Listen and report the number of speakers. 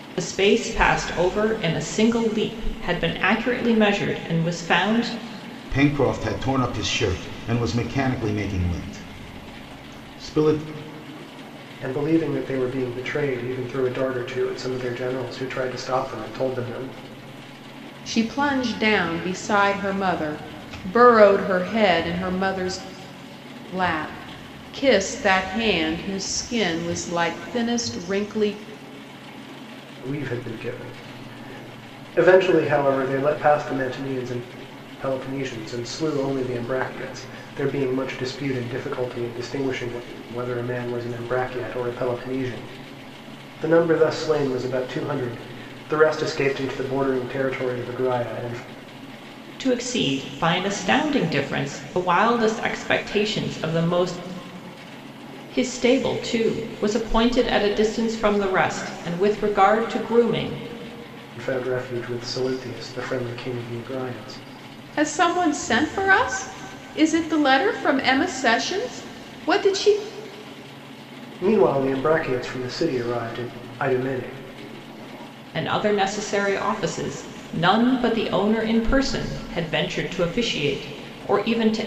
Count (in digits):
4